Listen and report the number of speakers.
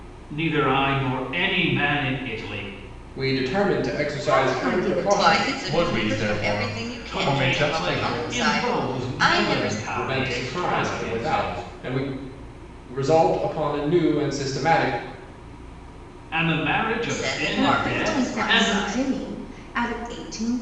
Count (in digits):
5